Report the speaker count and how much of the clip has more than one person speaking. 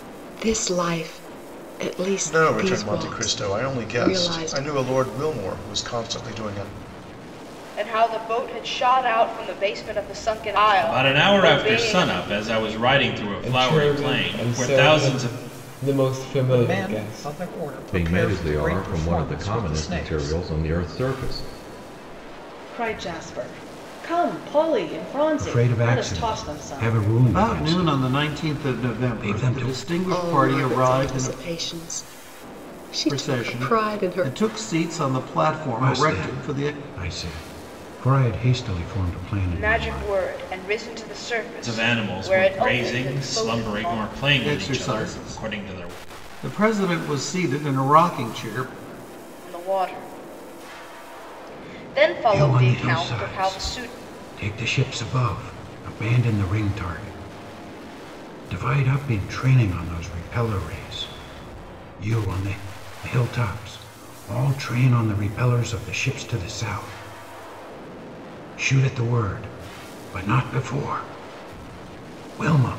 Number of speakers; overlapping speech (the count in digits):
10, about 32%